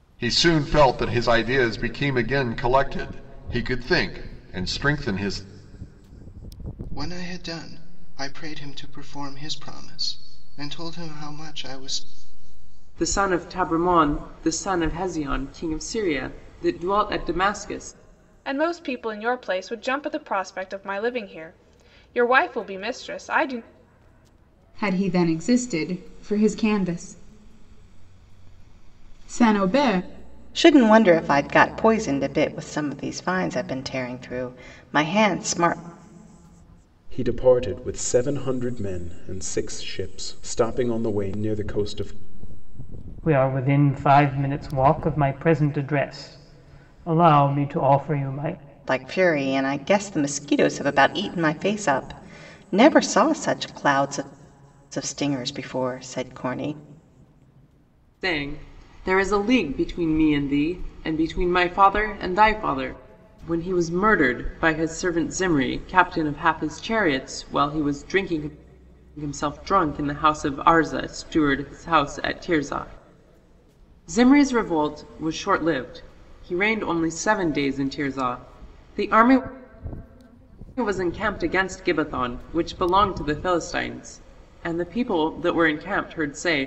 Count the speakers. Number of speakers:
8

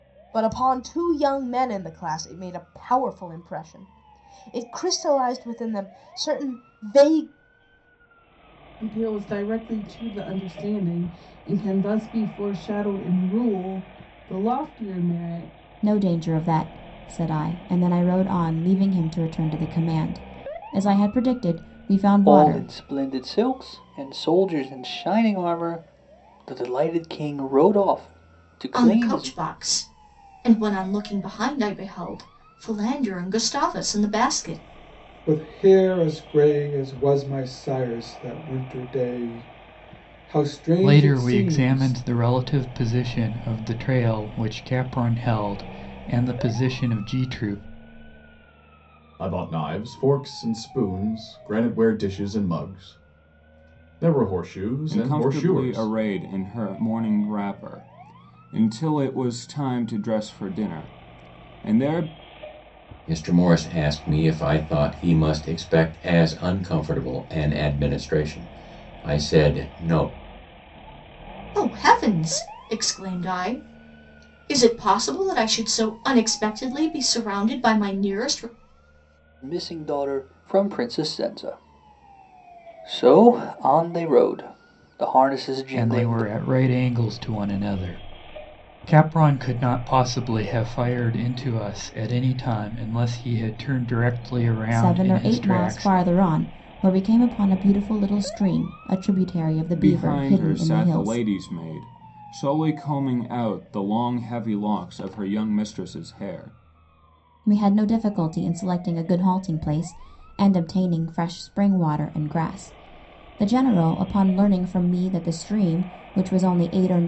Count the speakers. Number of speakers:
10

